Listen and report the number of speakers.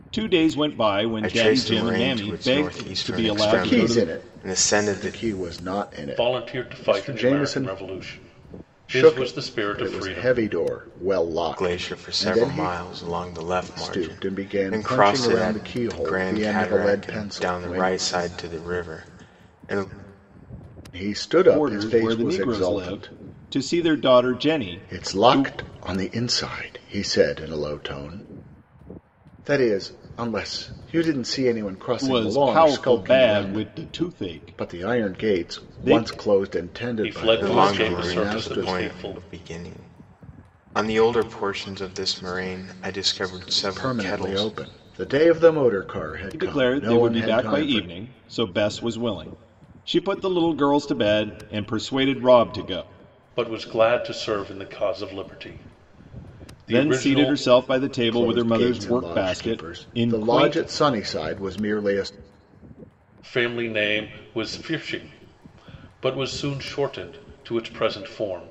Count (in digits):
4